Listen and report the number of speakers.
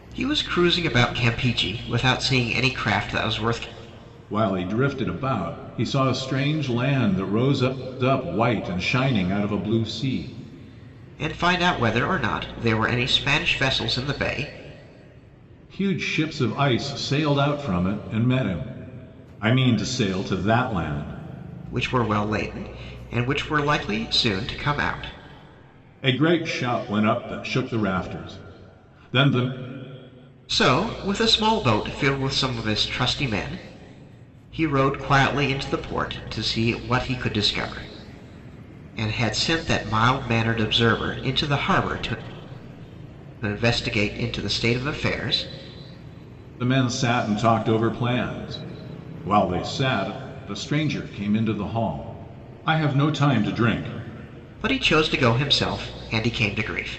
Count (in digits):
2